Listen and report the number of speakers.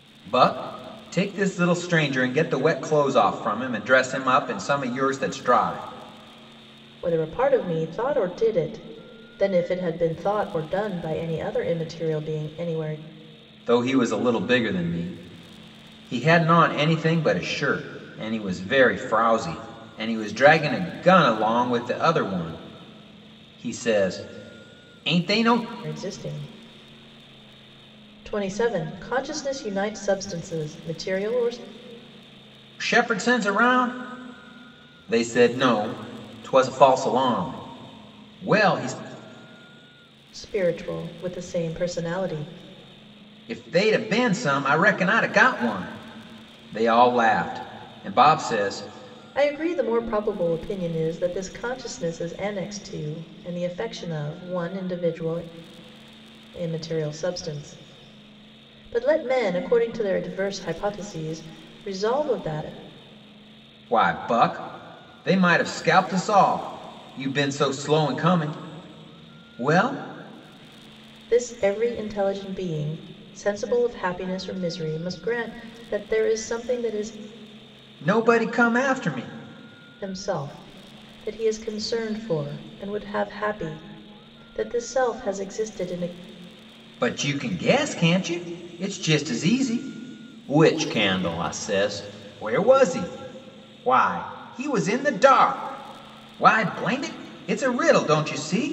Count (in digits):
2